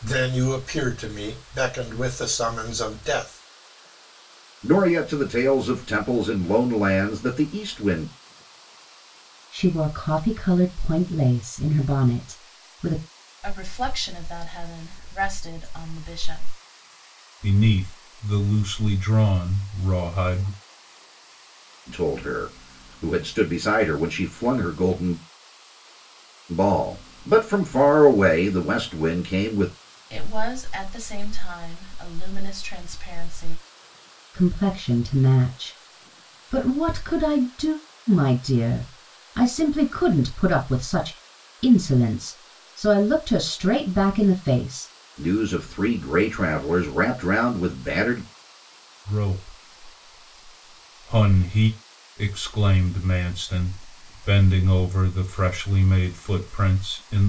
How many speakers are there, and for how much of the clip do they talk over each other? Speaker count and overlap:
5, no overlap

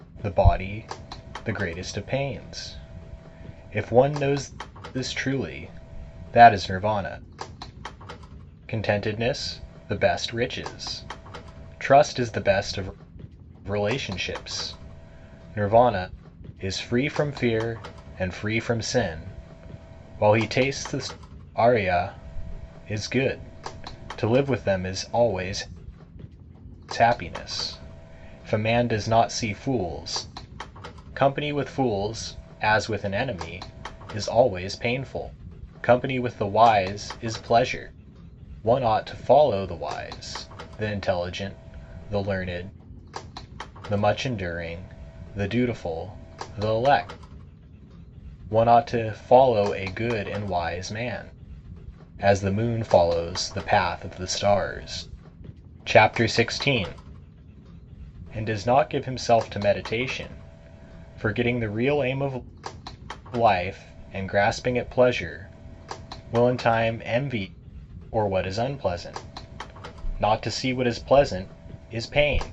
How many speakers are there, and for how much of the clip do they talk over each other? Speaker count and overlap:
1, no overlap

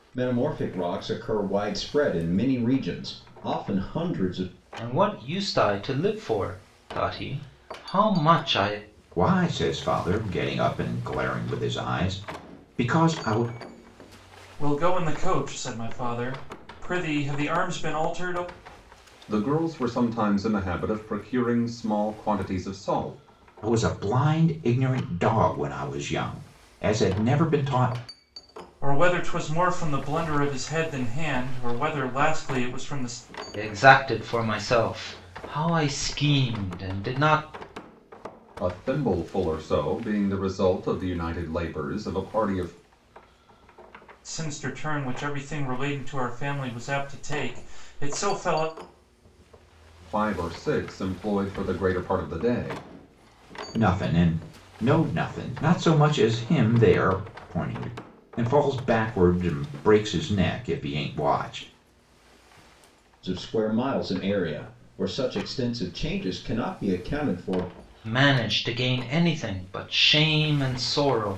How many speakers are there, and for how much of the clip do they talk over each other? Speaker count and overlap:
5, no overlap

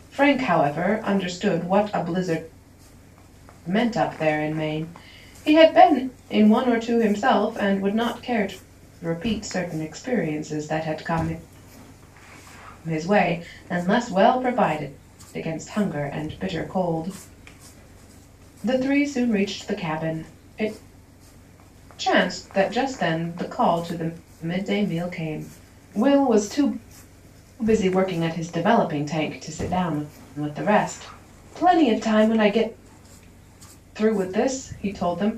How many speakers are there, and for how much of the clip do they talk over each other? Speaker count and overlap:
1, no overlap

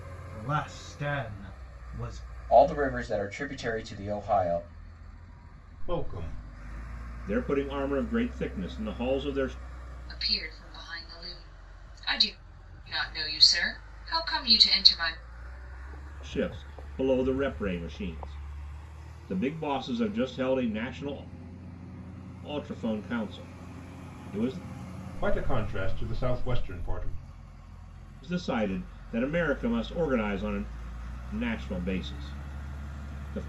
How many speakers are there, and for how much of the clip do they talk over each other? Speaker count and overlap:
5, no overlap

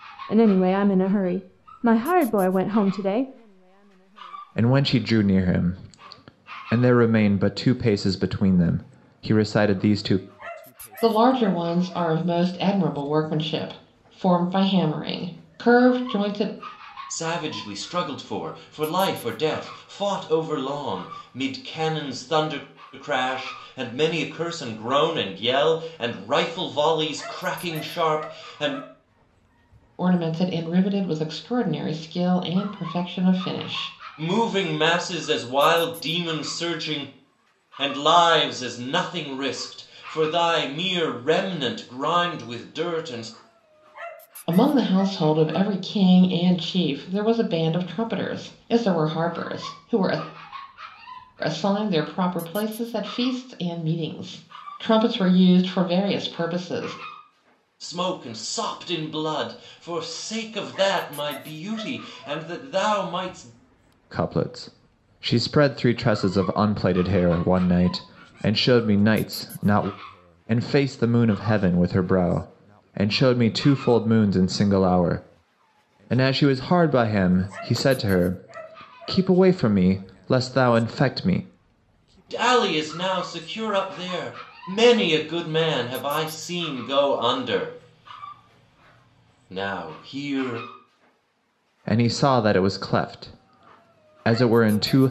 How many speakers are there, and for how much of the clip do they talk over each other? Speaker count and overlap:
4, no overlap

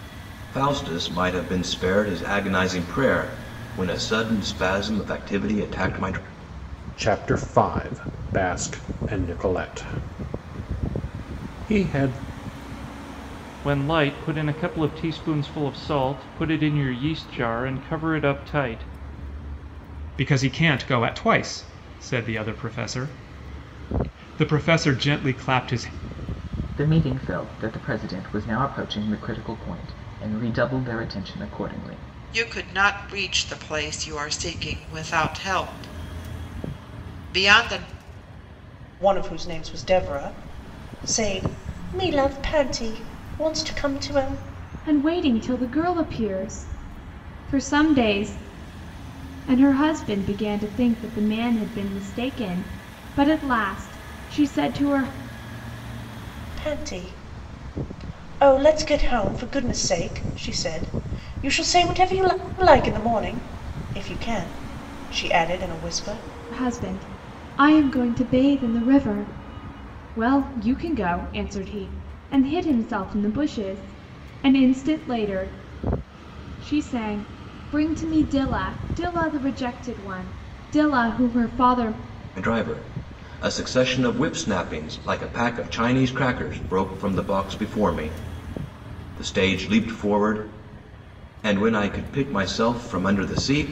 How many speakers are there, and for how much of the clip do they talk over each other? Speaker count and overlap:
8, no overlap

